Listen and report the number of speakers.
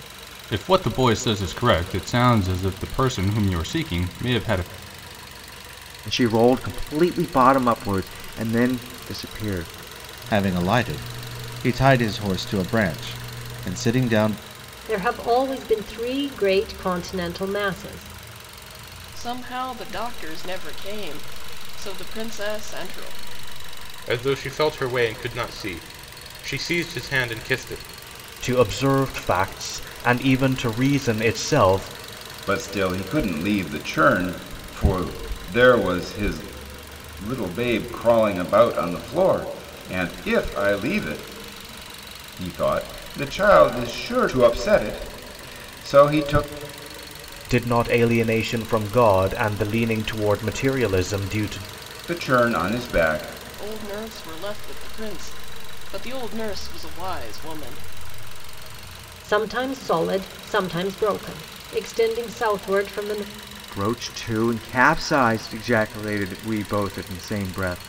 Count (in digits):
8